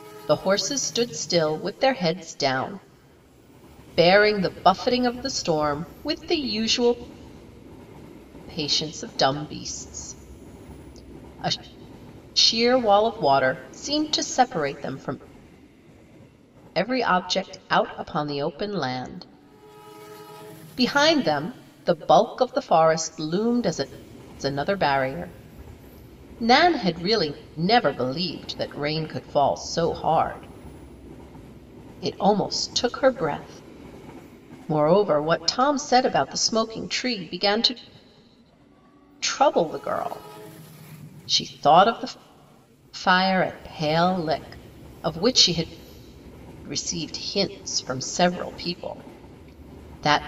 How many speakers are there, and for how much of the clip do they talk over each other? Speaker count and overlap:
1, no overlap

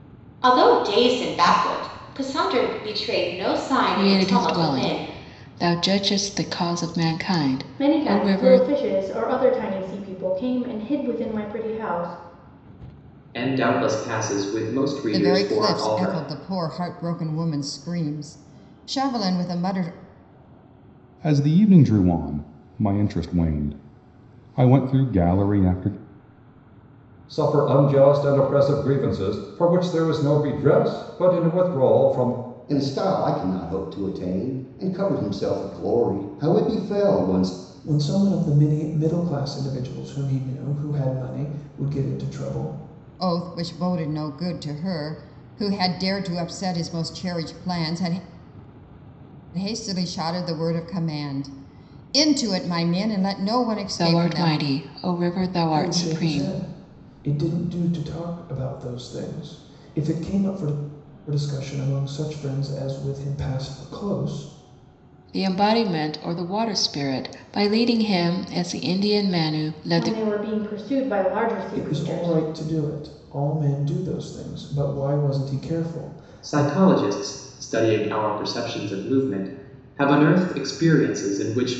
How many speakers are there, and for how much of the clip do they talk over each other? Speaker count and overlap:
9, about 8%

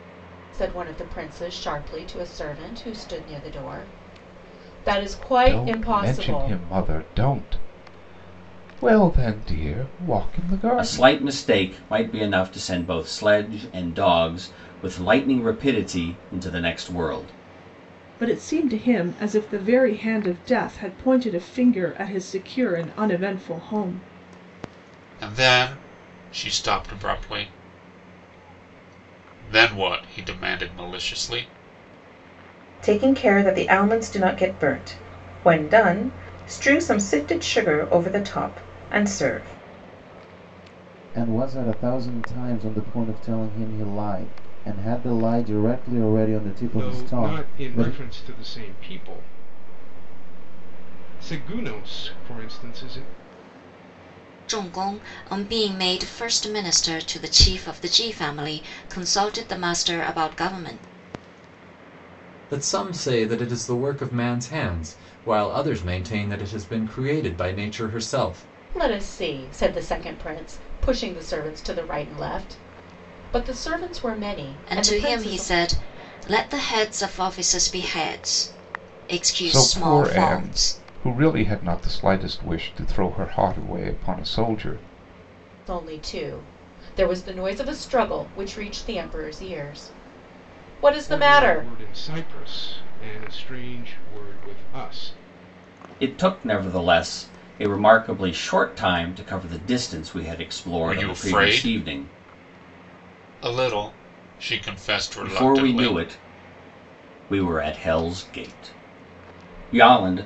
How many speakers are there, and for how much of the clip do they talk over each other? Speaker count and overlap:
10, about 7%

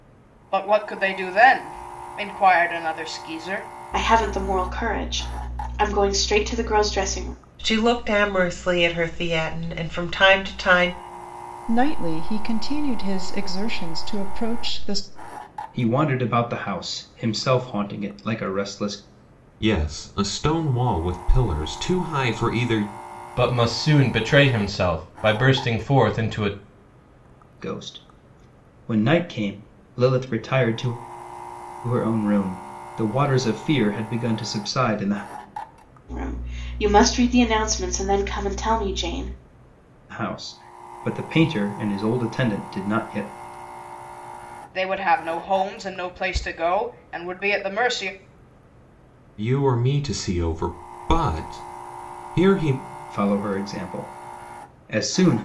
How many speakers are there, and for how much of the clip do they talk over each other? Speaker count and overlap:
7, no overlap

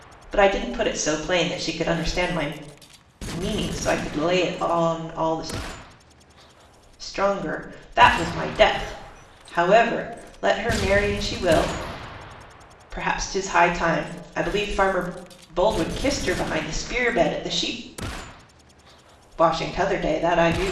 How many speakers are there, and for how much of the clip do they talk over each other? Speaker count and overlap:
1, no overlap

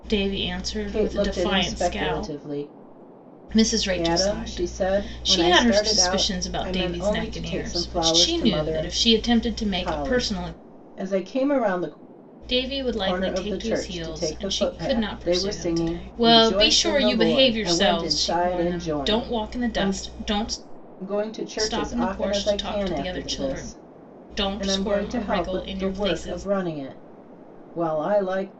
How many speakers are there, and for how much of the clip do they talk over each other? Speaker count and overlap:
2, about 65%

